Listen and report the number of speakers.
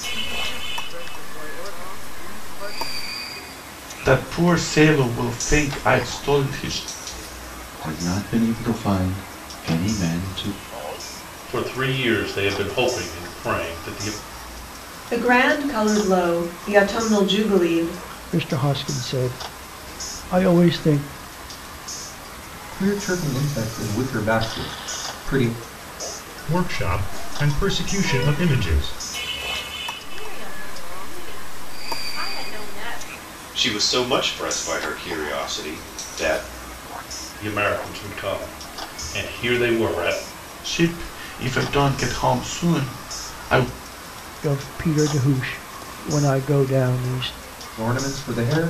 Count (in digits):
10